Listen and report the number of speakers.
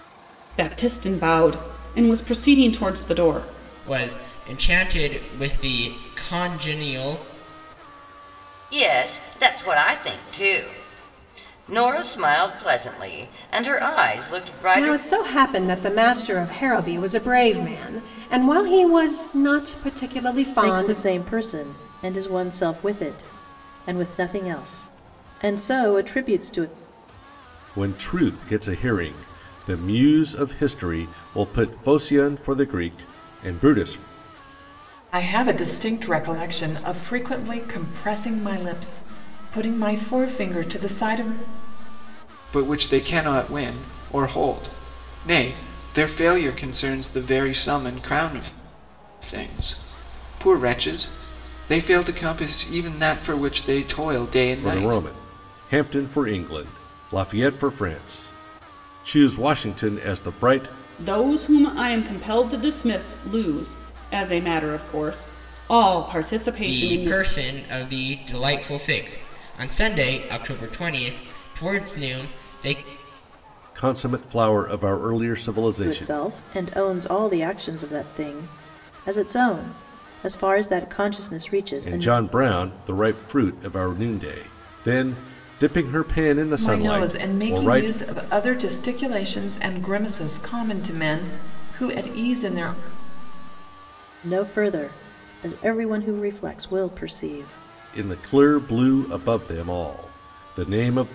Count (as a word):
eight